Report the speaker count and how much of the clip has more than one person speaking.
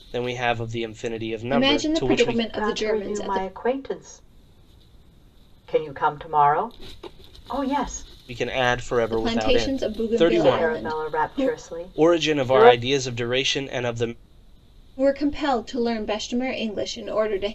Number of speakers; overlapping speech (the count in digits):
3, about 30%